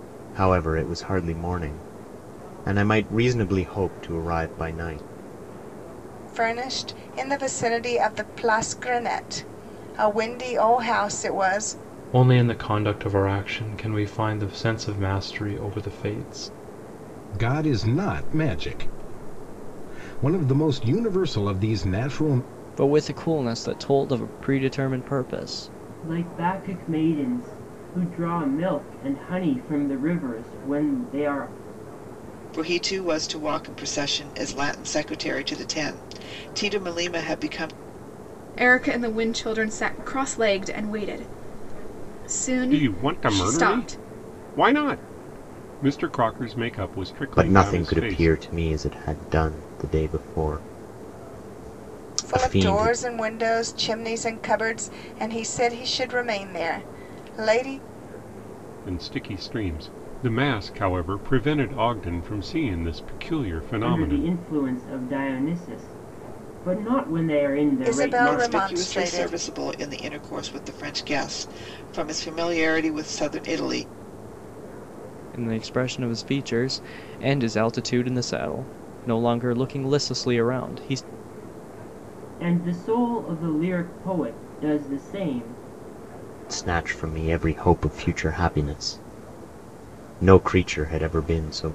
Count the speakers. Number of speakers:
9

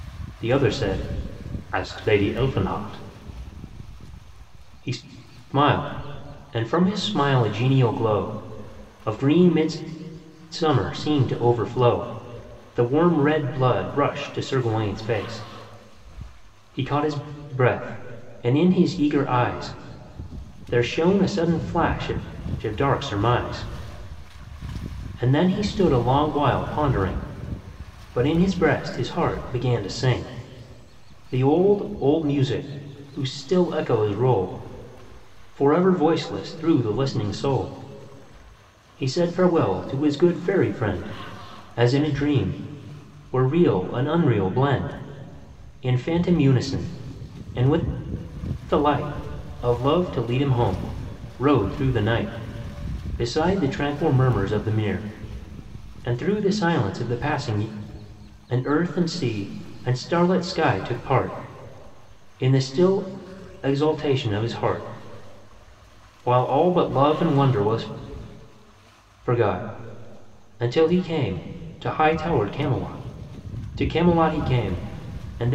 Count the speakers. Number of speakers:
1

